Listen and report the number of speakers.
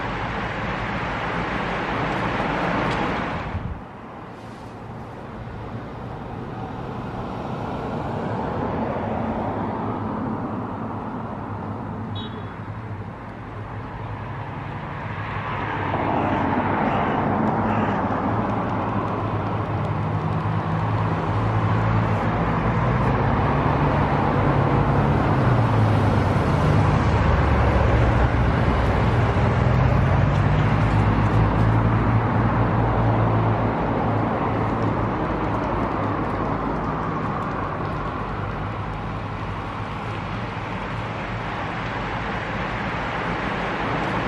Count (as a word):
zero